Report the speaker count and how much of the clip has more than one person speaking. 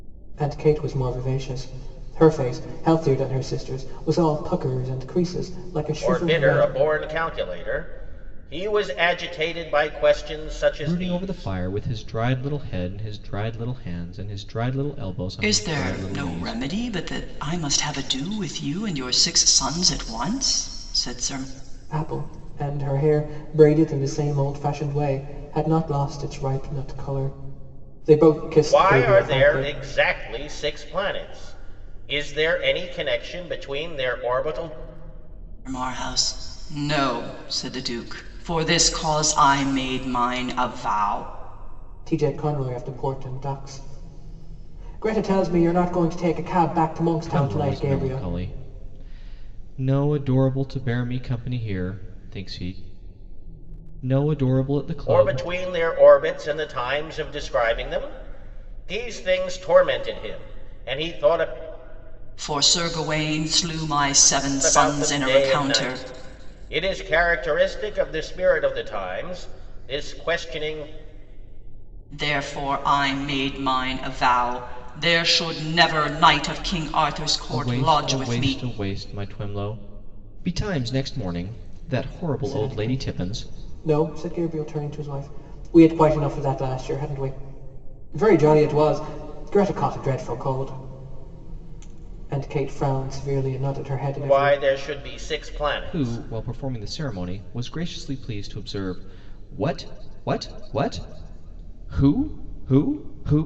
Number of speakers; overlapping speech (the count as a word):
four, about 9%